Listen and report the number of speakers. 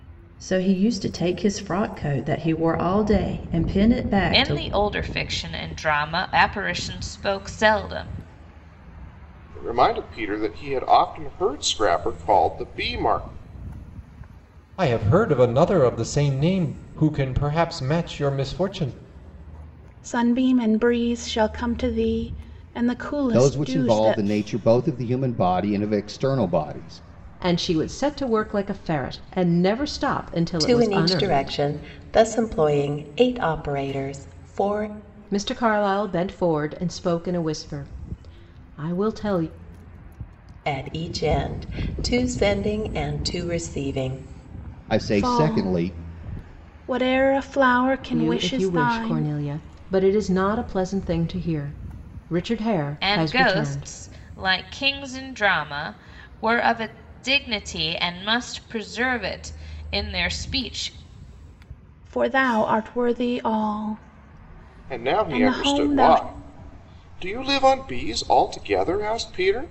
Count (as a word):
eight